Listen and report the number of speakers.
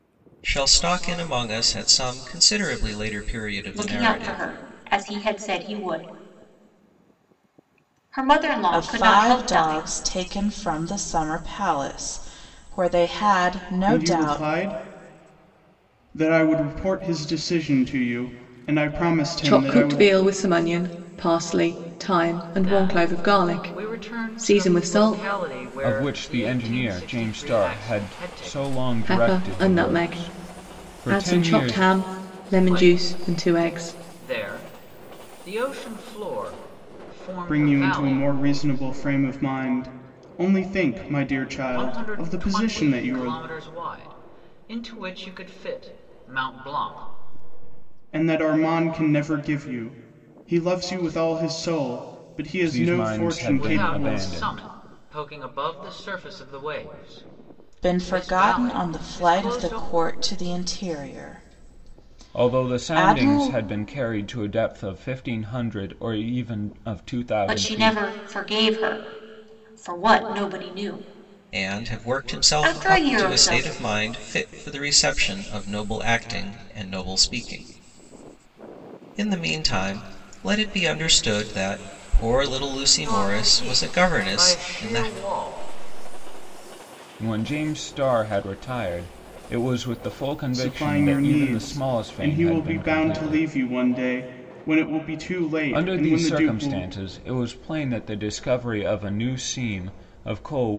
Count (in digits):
7